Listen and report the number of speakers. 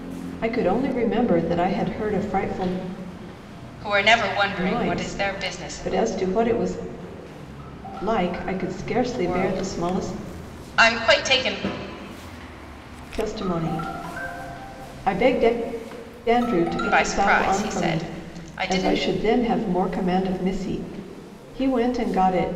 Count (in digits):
2